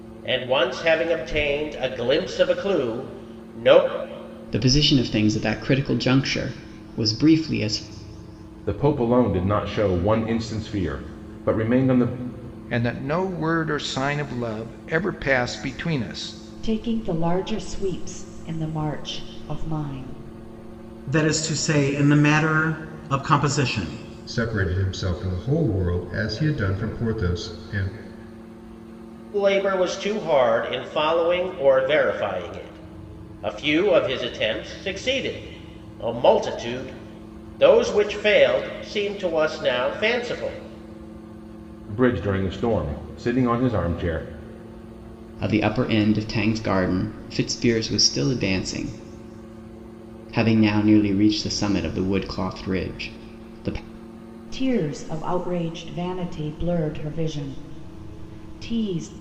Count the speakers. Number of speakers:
7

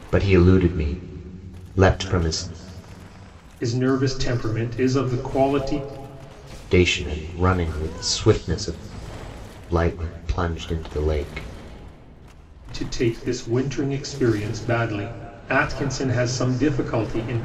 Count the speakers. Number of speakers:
2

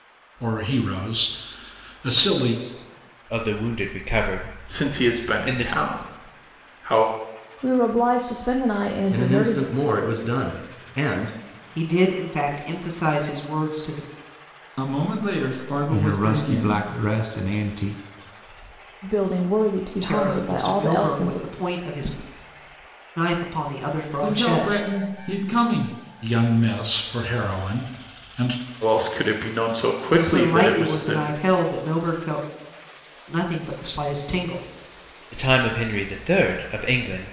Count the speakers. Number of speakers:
8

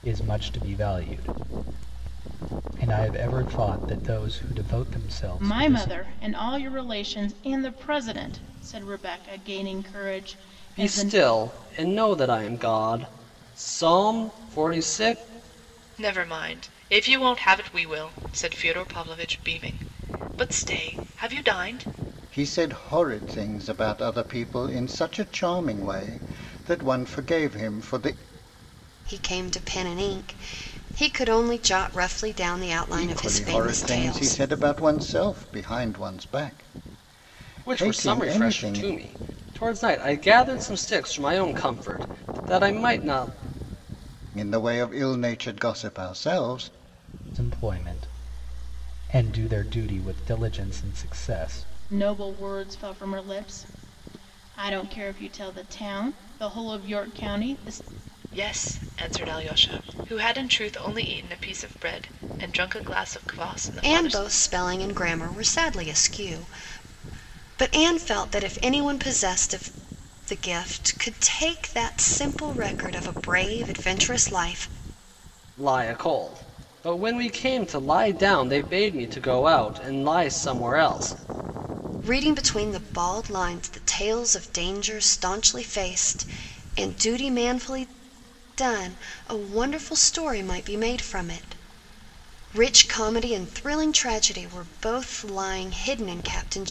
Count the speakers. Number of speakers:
6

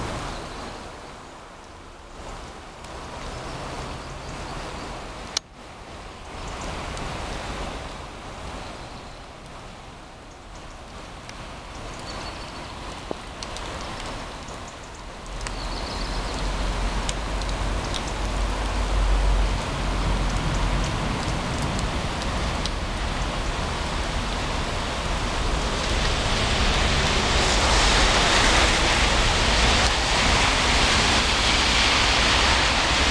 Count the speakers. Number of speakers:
0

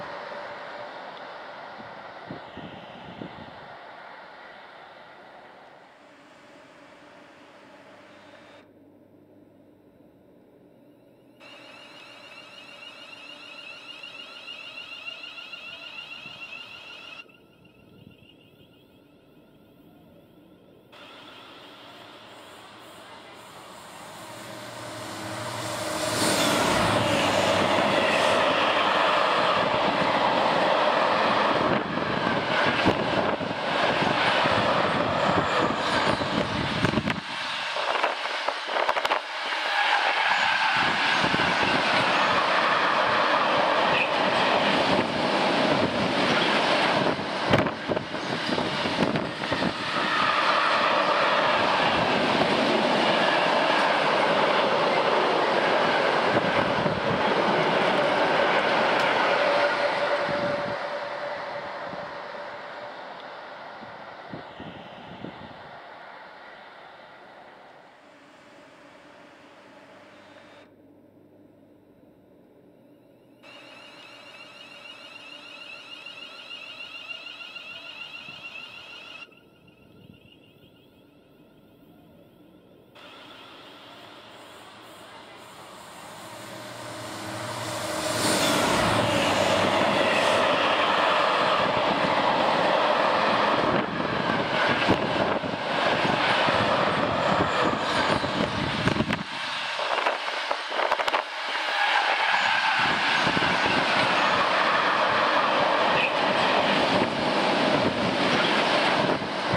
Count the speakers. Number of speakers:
0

